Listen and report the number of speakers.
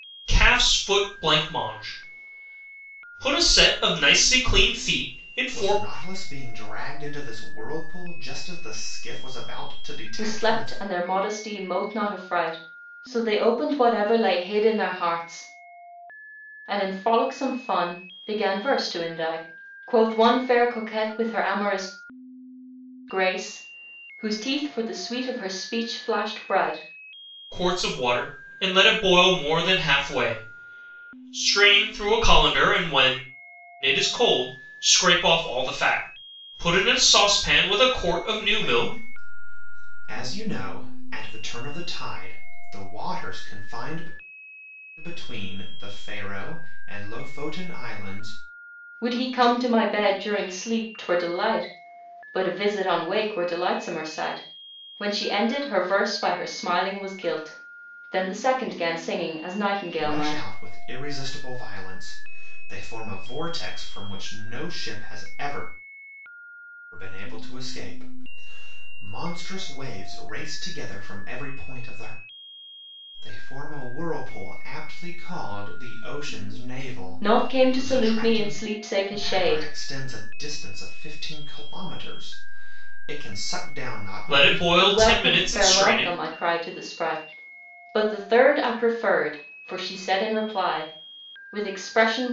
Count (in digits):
3